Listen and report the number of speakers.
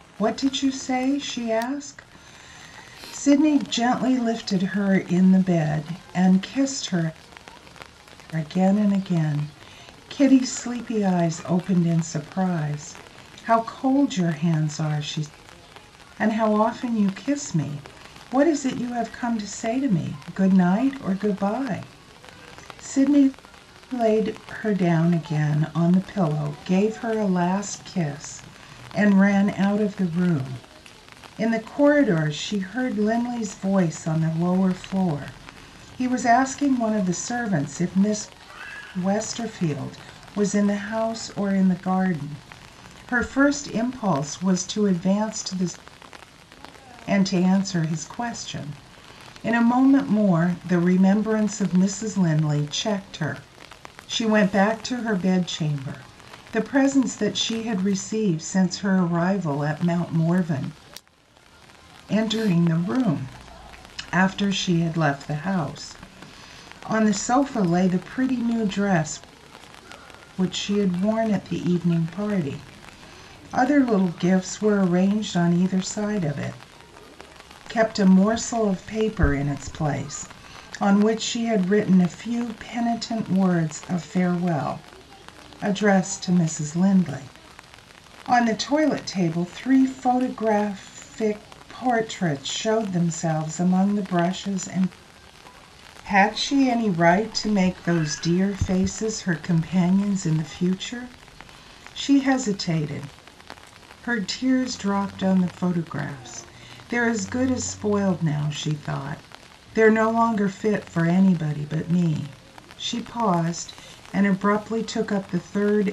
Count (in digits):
1